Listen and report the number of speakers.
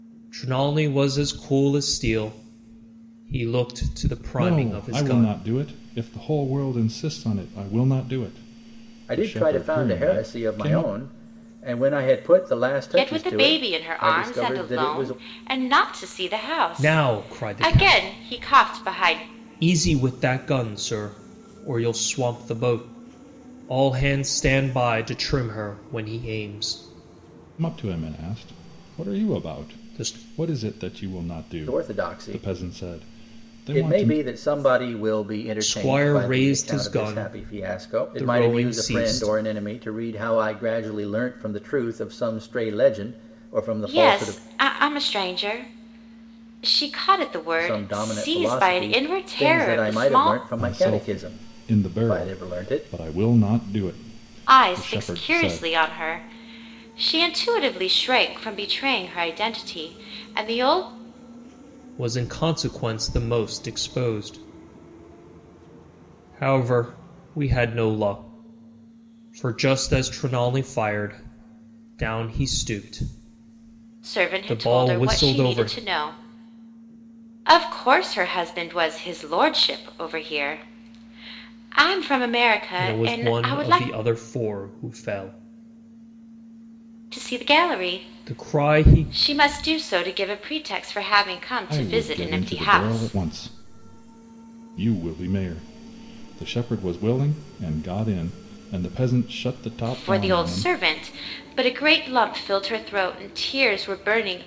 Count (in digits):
4